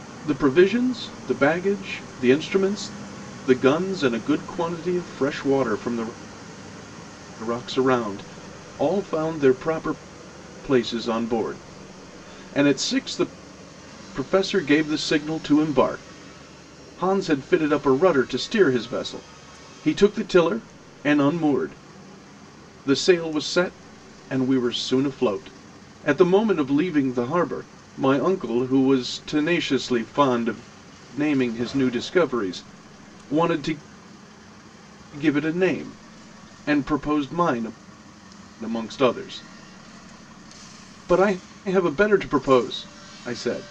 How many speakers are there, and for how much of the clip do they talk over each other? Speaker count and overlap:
one, no overlap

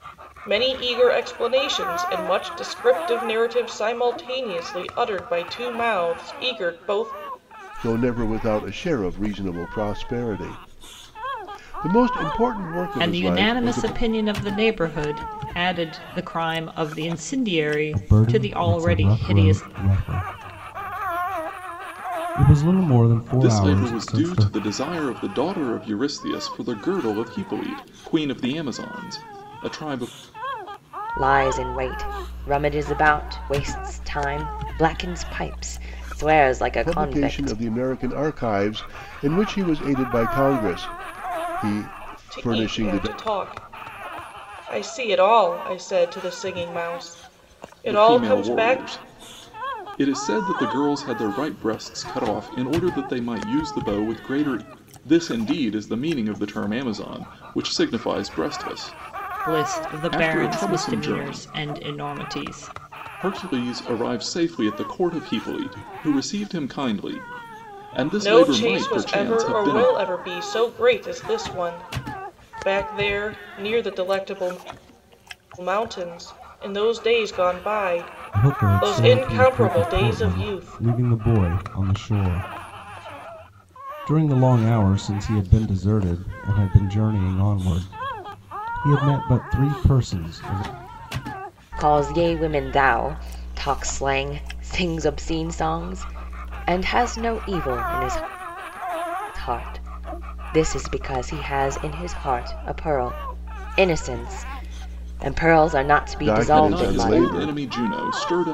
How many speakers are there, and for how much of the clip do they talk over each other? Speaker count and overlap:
six, about 13%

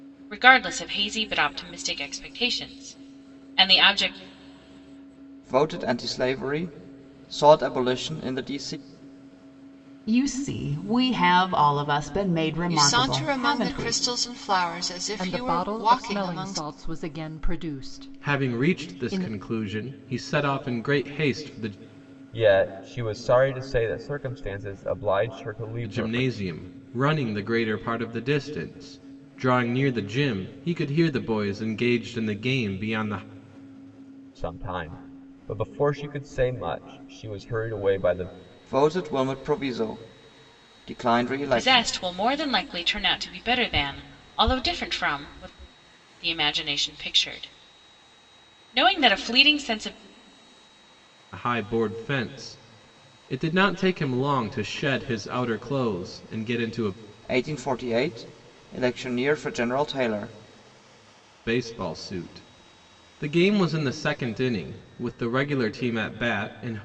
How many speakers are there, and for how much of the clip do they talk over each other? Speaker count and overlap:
seven, about 9%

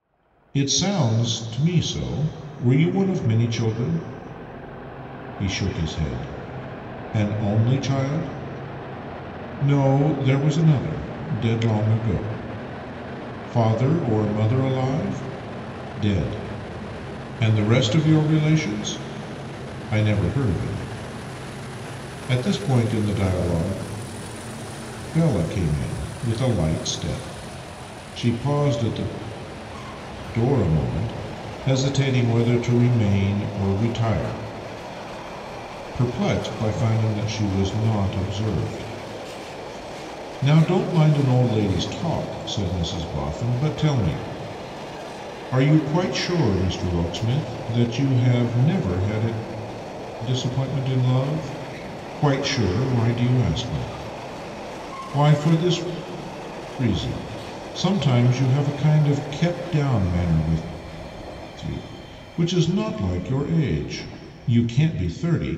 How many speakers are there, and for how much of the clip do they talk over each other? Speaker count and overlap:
one, no overlap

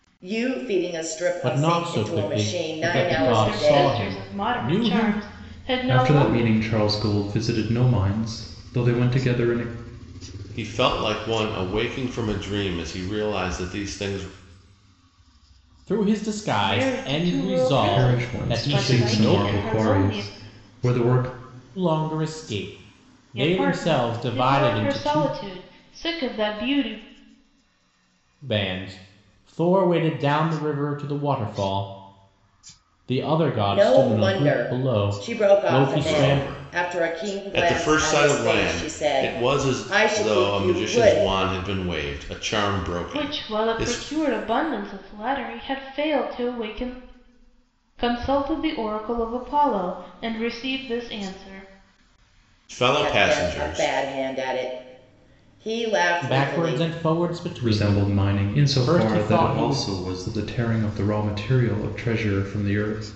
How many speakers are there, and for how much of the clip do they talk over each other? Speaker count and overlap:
five, about 35%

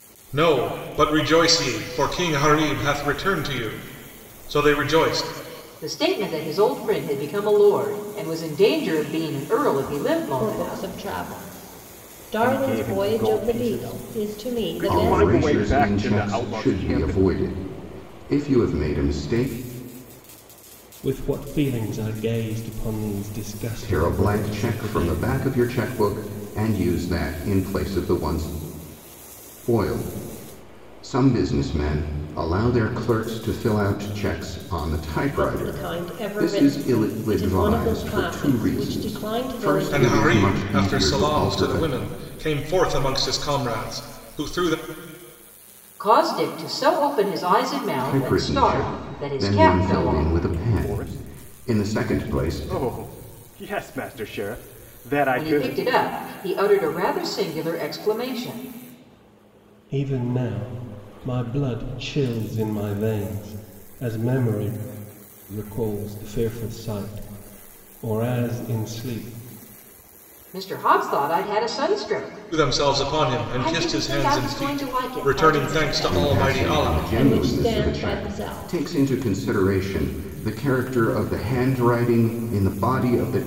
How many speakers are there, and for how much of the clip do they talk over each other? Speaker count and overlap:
six, about 30%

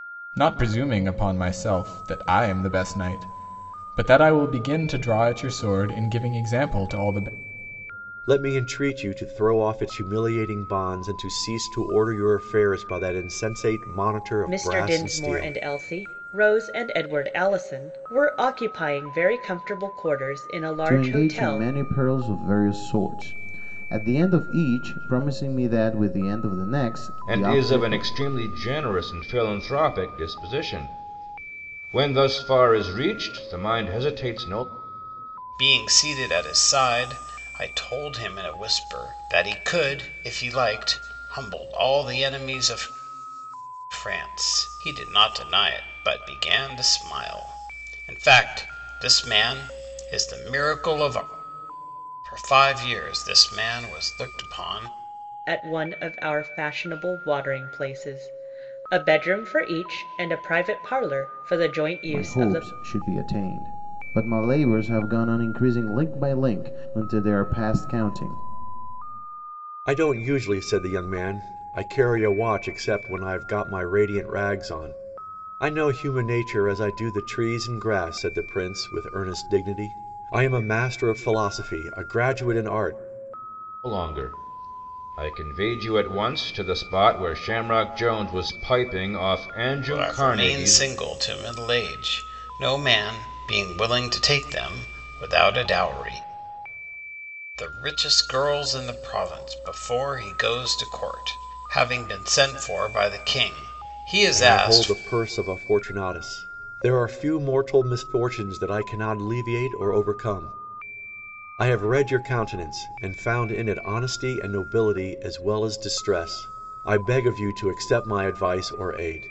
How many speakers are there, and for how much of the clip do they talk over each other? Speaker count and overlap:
six, about 4%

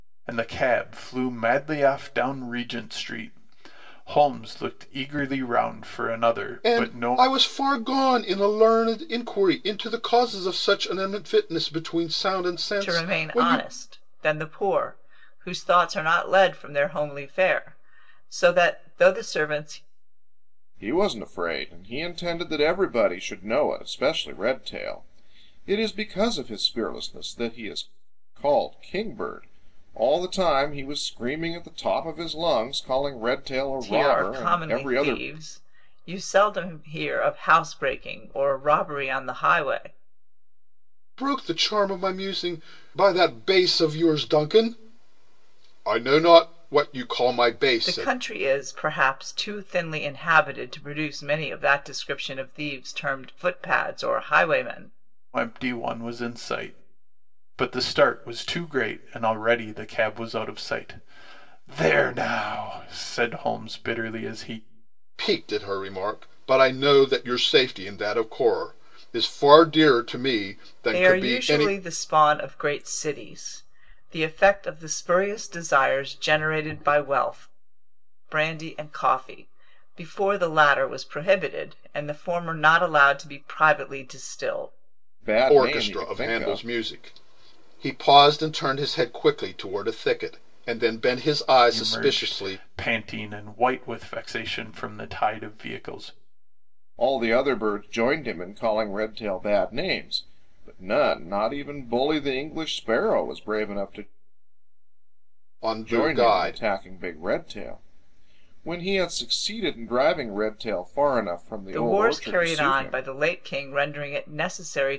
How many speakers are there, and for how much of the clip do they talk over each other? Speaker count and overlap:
four, about 7%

